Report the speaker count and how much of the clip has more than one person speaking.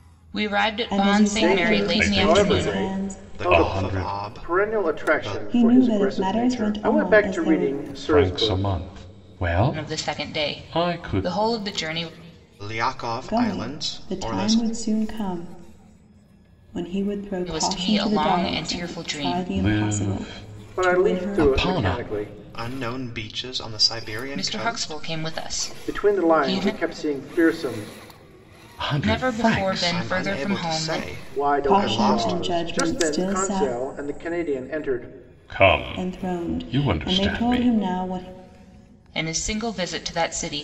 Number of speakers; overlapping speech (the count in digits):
5, about 57%